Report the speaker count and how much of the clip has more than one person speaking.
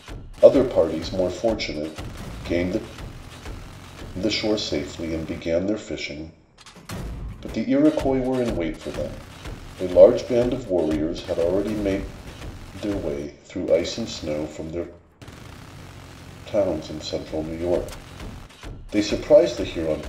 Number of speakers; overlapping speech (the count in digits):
1, no overlap